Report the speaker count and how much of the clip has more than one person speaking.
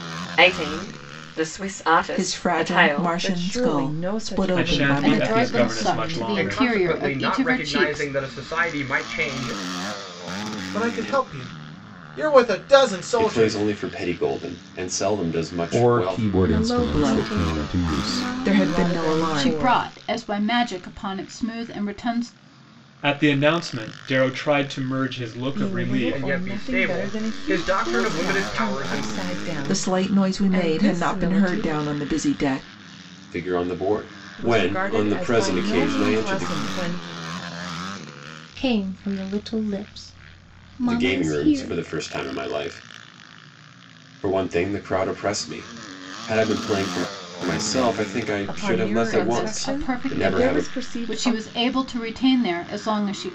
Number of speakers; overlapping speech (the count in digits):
10, about 42%